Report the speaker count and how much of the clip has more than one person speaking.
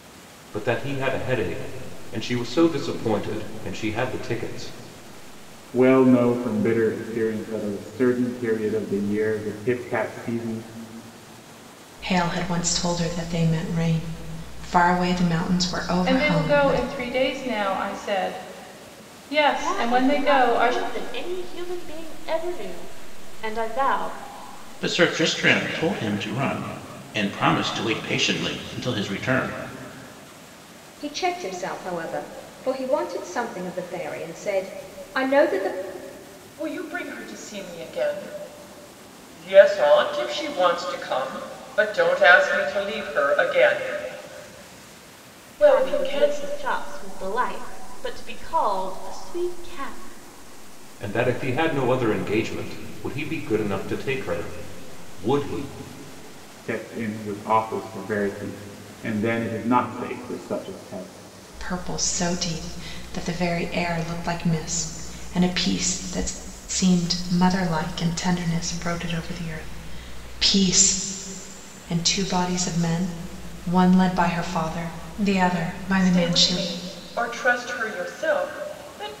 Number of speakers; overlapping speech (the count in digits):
8, about 5%